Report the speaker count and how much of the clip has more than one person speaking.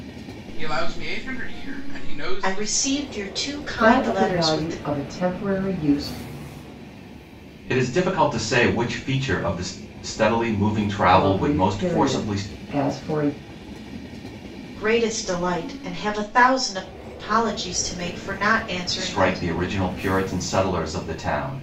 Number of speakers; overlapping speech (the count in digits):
4, about 16%